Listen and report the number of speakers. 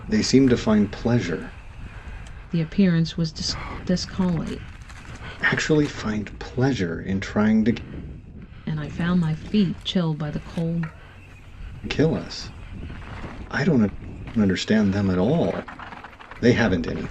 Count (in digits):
2